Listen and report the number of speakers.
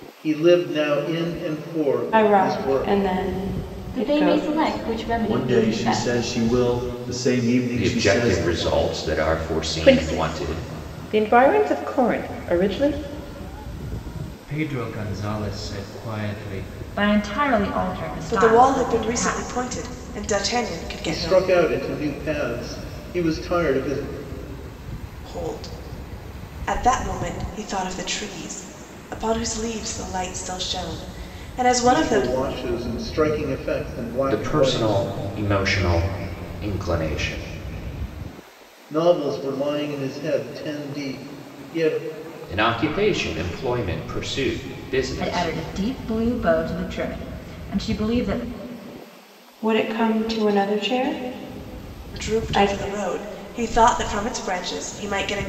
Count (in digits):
9